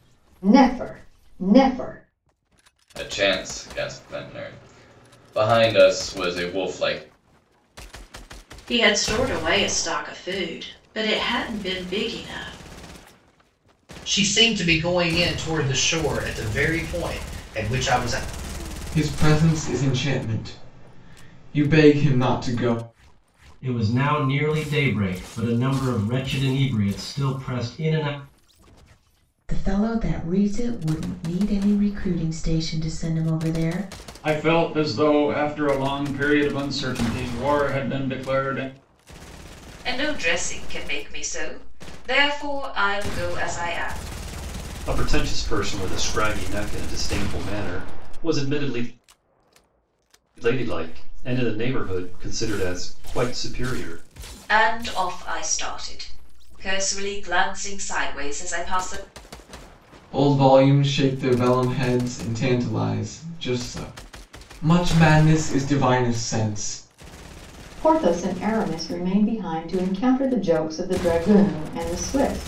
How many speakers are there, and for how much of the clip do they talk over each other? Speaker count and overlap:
10, no overlap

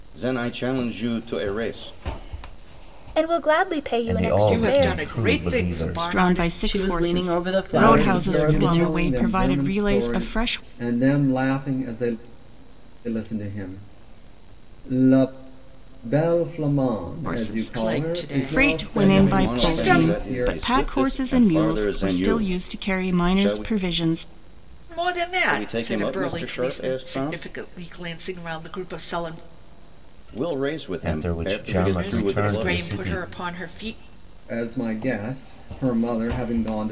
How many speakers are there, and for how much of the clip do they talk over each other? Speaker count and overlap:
7, about 47%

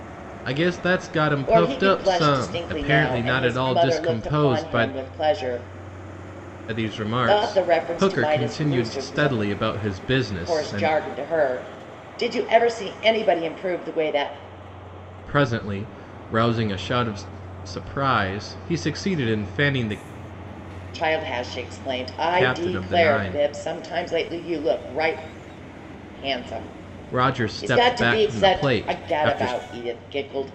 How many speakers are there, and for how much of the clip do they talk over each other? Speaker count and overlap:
2, about 33%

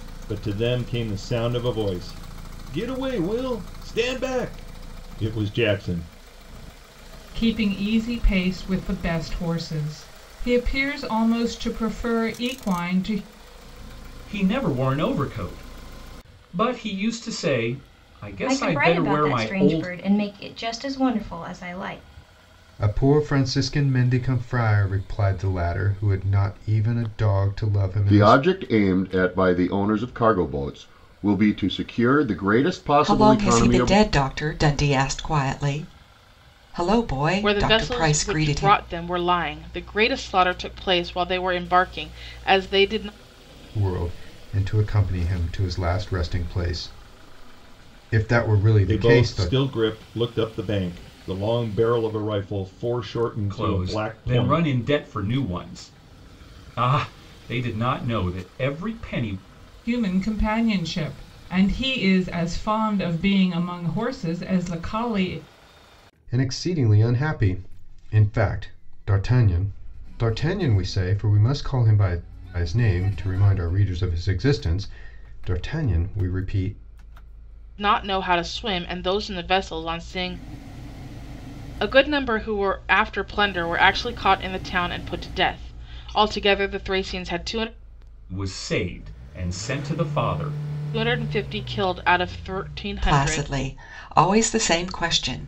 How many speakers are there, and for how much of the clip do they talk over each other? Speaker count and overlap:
8, about 7%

